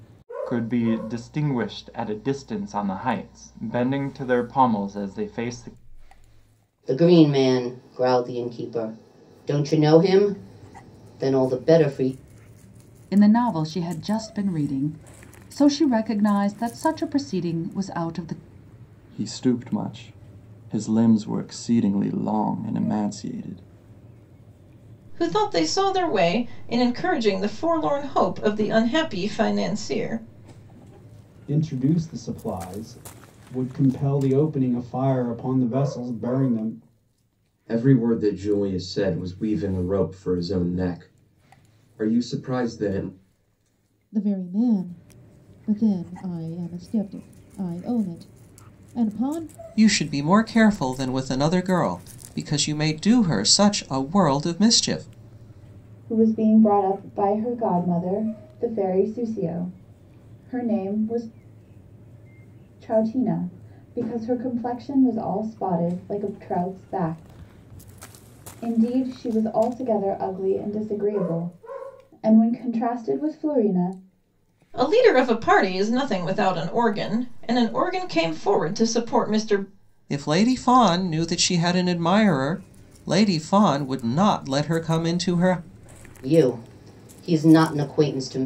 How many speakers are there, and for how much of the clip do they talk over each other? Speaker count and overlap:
10, no overlap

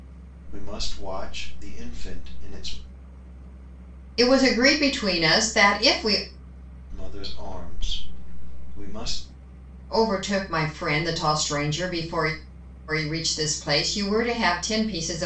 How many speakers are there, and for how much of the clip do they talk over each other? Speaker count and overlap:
2, no overlap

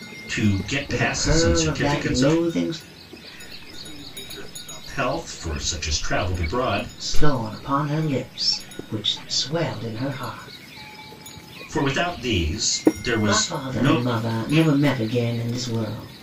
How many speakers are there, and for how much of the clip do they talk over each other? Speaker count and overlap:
3, about 47%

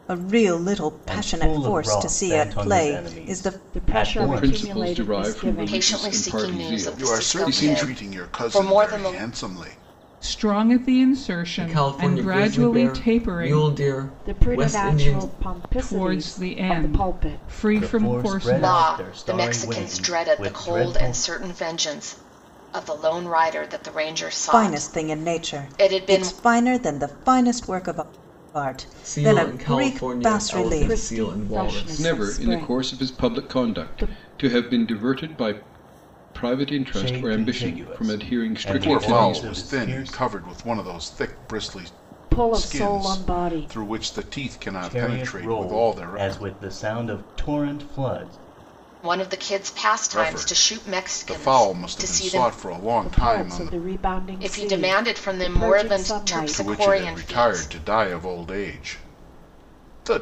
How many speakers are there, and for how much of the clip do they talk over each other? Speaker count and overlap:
8, about 60%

